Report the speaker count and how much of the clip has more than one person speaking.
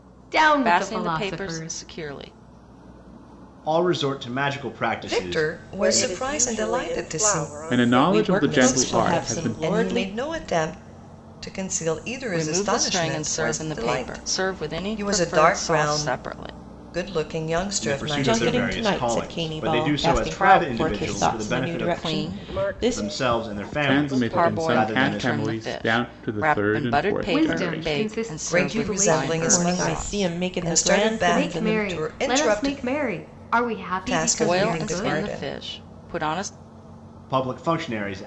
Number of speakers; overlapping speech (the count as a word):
seven, about 69%